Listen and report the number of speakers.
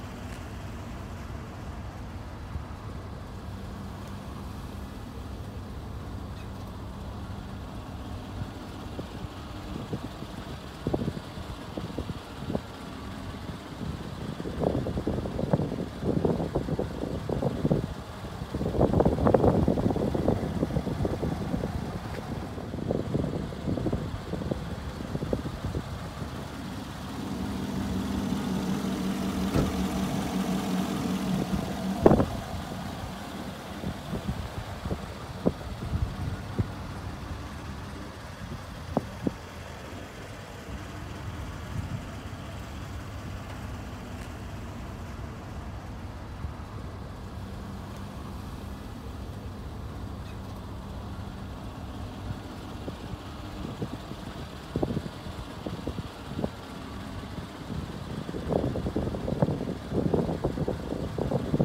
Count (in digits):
0